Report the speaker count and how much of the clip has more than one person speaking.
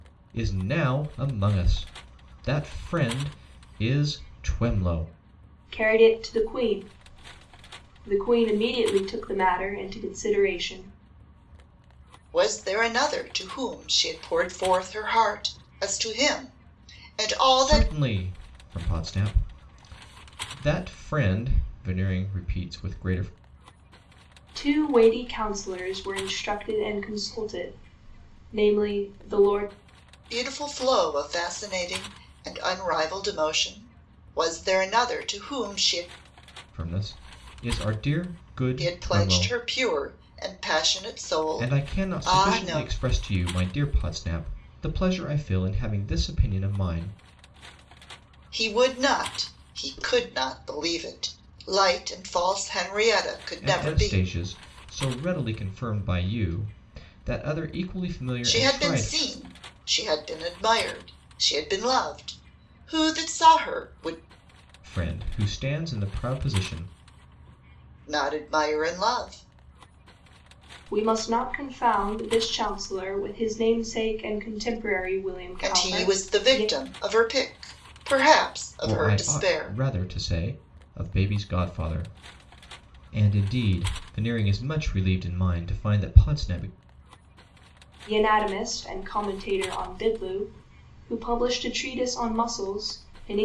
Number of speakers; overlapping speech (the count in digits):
3, about 6%